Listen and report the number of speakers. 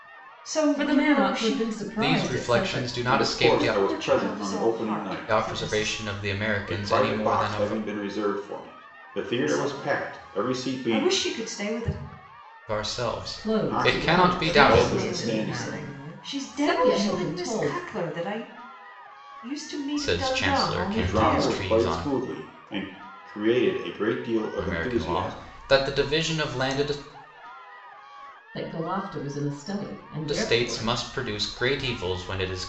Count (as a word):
four